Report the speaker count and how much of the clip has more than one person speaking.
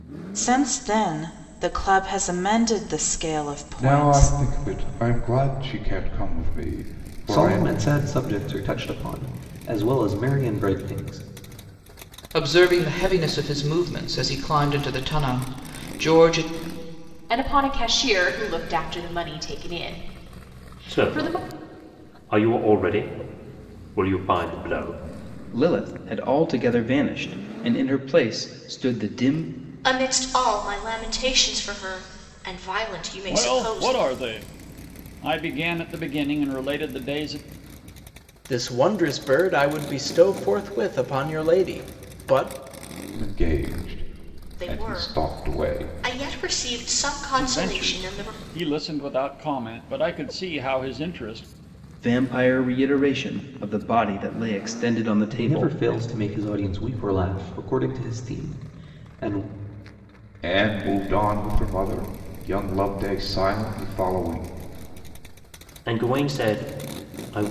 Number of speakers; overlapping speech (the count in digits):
10, about 8%